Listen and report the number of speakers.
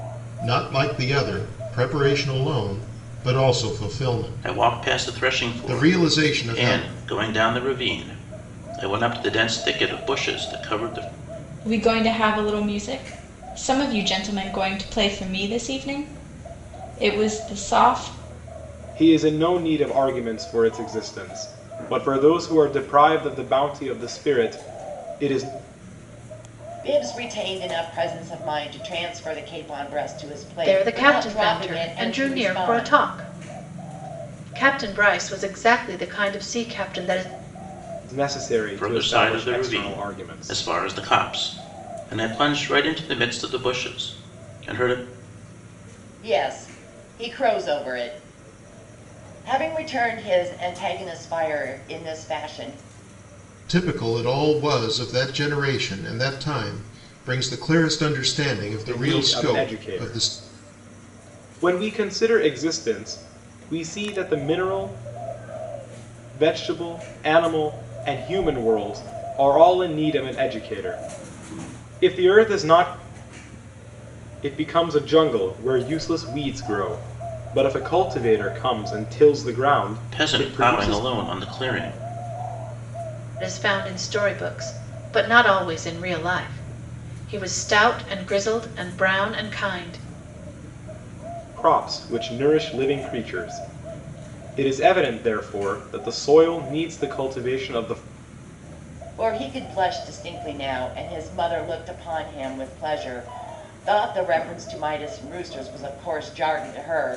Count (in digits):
6